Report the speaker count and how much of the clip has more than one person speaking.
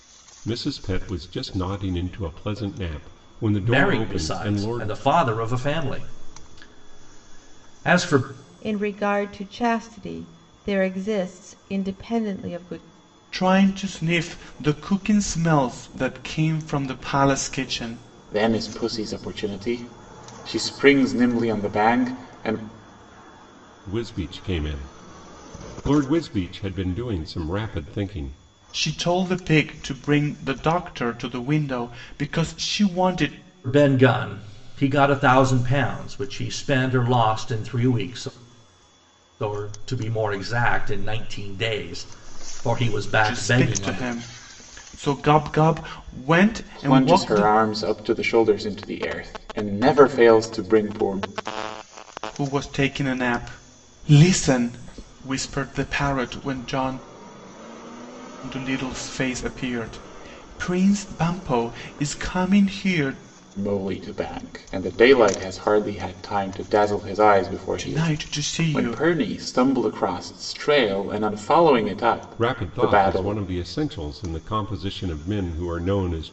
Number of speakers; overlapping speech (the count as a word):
five, about 6%